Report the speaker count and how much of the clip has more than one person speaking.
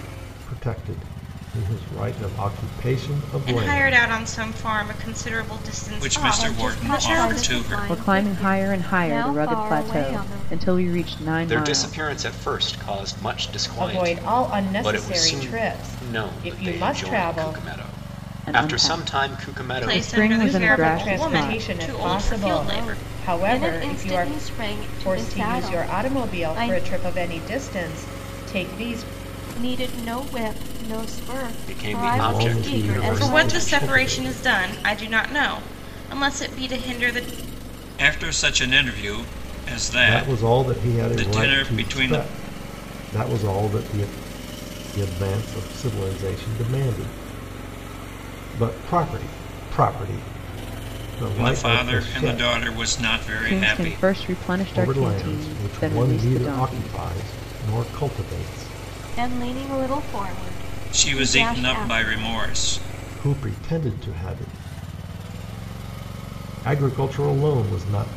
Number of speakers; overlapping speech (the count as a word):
seven, about 40%